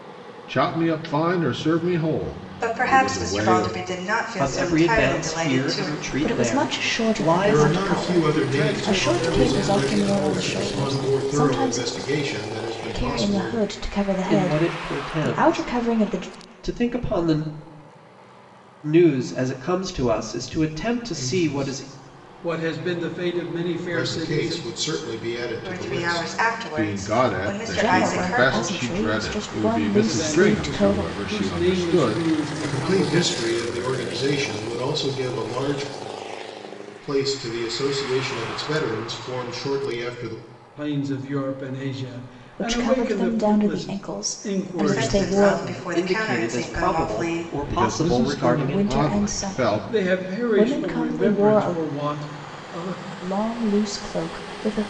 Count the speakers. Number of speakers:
six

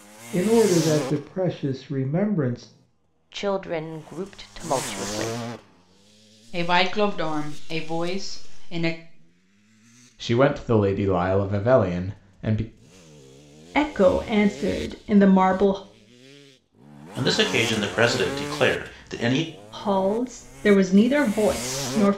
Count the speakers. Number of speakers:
six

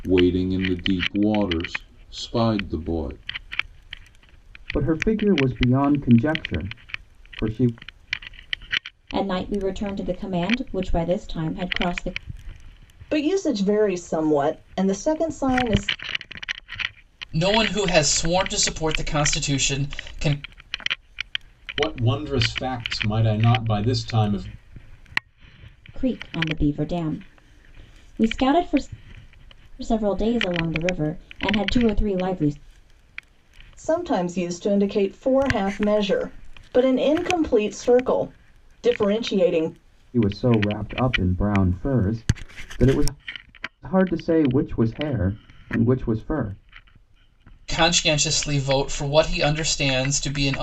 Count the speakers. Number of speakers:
six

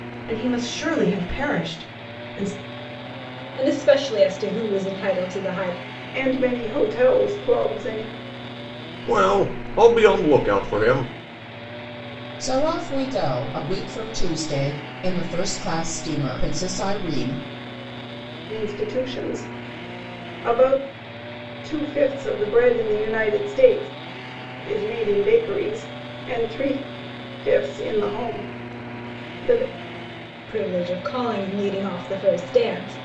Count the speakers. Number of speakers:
five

